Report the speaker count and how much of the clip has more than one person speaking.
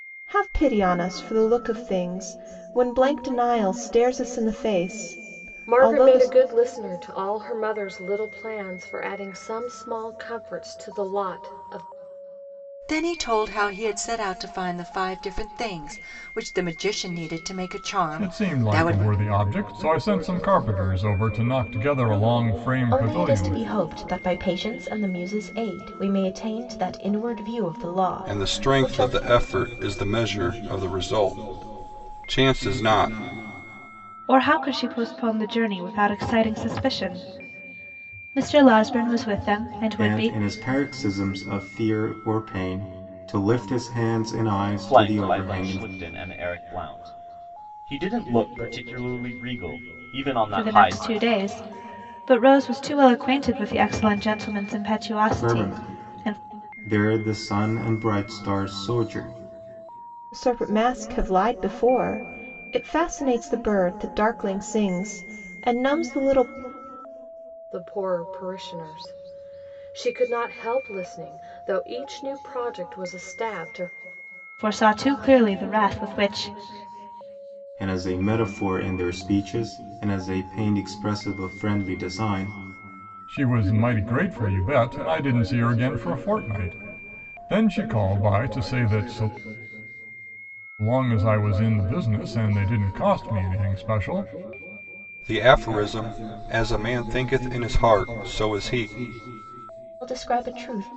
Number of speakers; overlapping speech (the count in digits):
9, about 6%